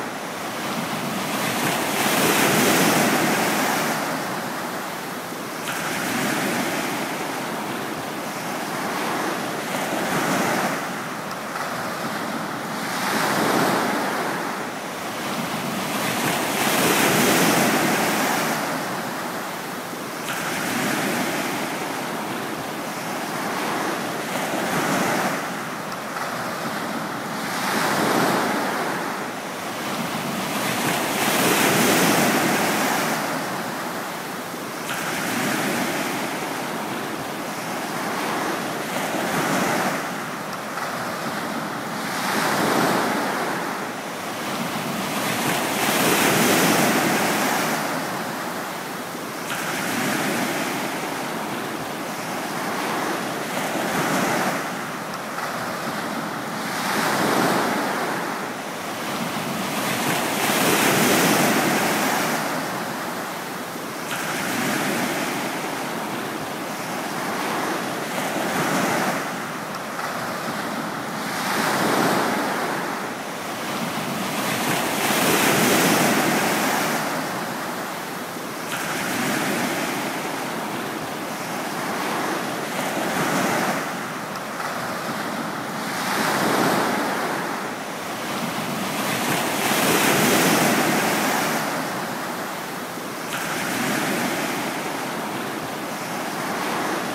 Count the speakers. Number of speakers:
zero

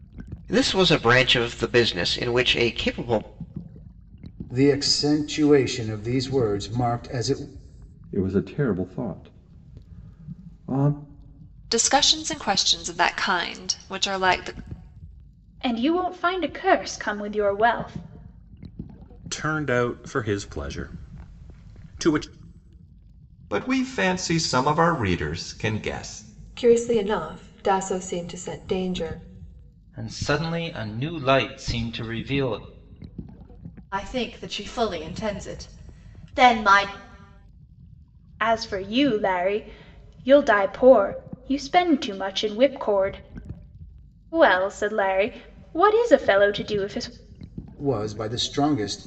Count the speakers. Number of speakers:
ten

